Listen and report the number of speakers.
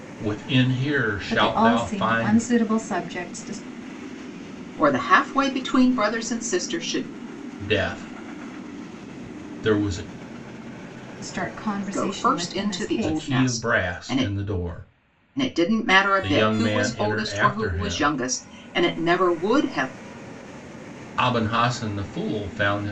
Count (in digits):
3